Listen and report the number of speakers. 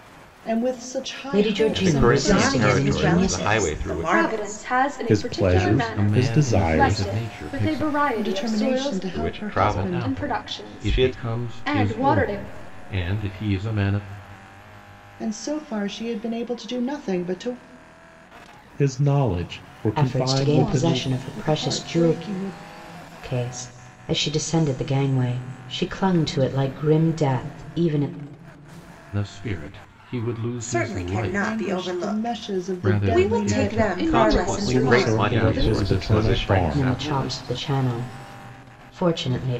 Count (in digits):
7